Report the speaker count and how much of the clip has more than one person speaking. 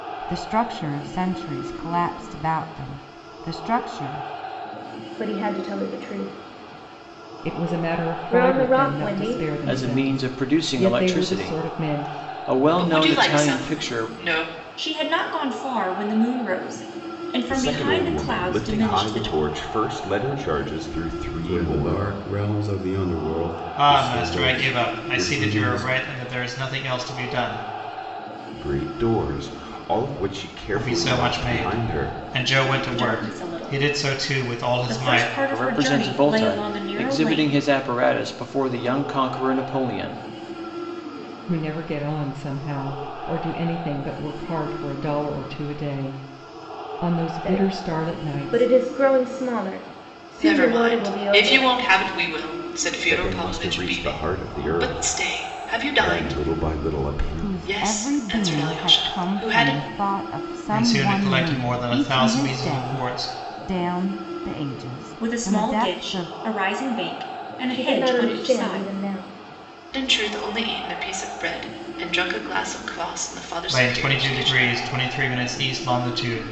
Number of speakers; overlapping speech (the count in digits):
9, about 43%